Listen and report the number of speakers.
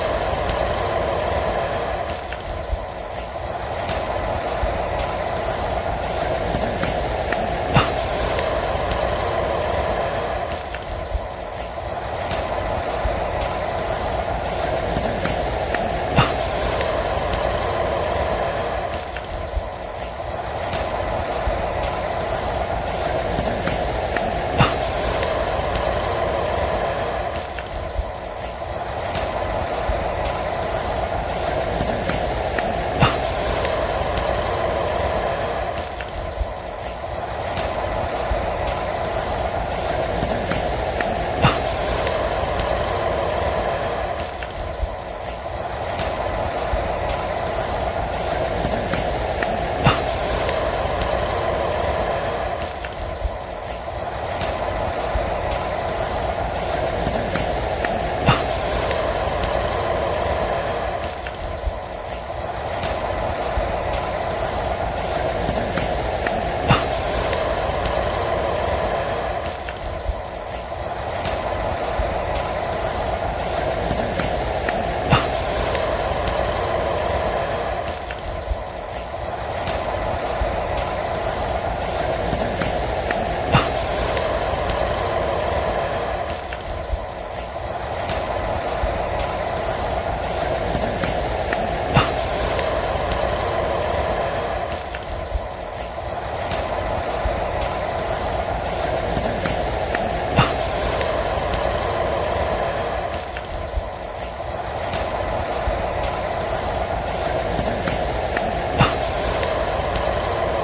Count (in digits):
0